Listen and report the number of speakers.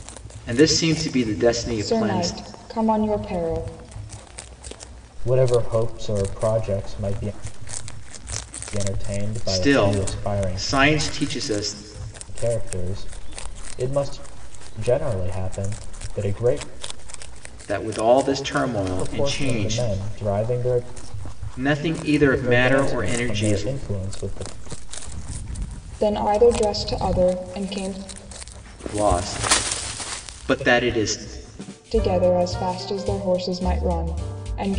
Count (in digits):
3